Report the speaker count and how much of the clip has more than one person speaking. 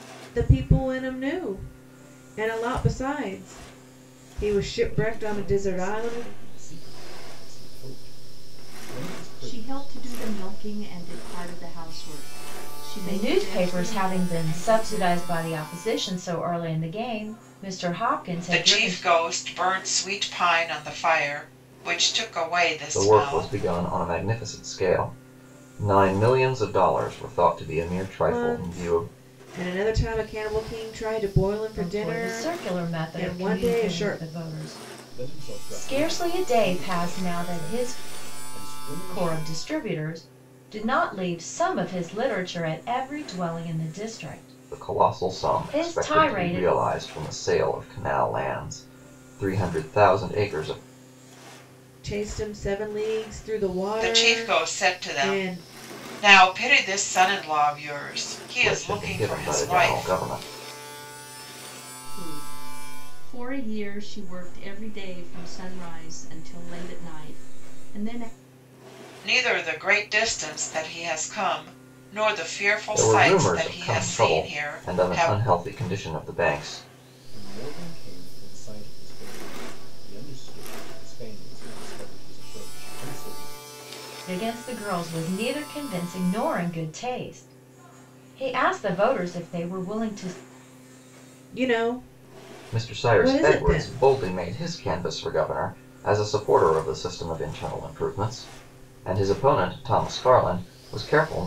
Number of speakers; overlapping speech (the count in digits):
6, about 22%